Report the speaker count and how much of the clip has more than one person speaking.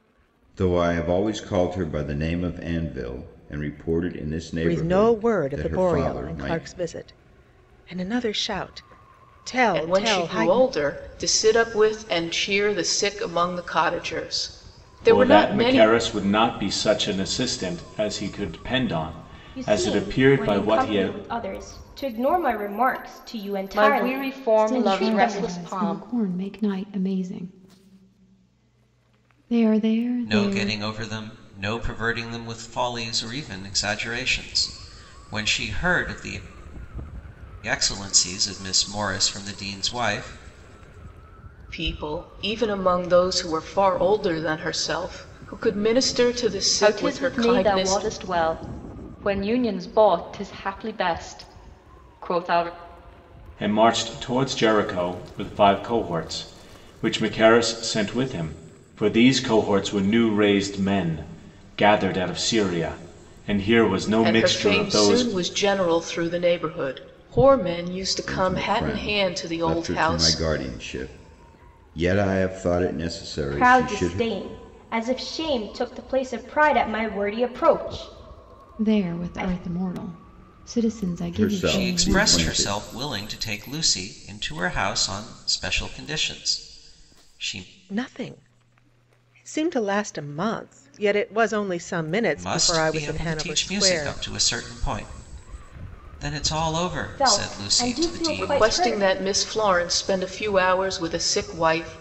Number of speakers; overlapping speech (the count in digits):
8, about 20%